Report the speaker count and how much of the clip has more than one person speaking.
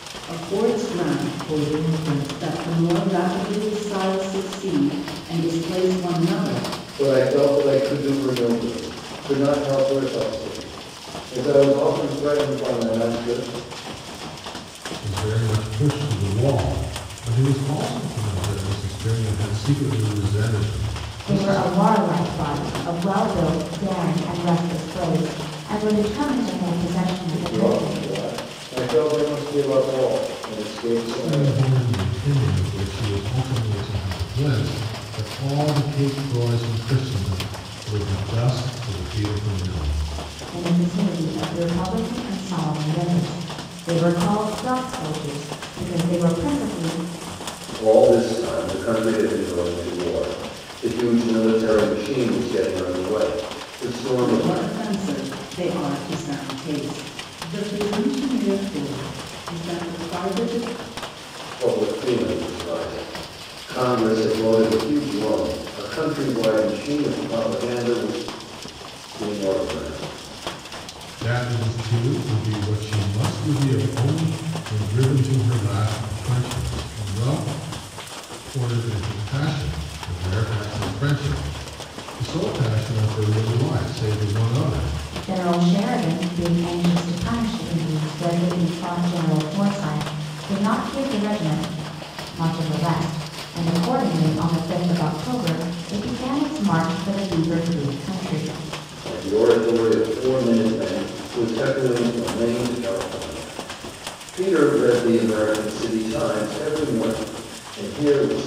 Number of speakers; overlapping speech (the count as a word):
four, about 2%